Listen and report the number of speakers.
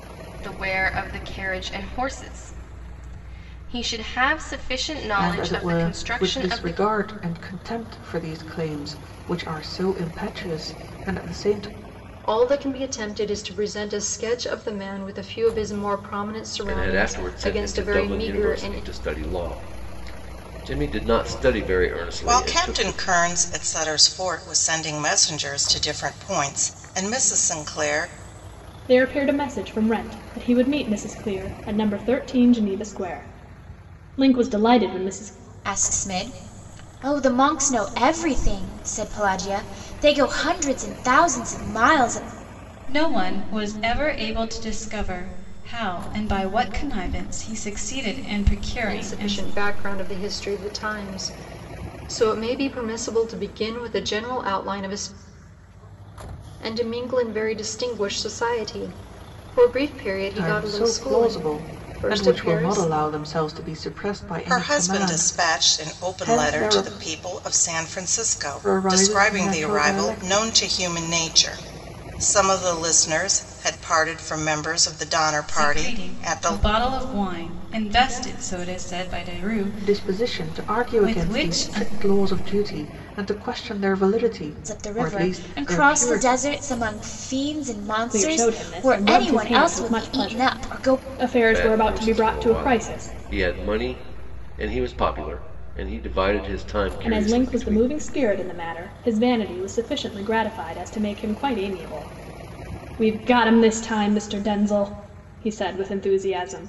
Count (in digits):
8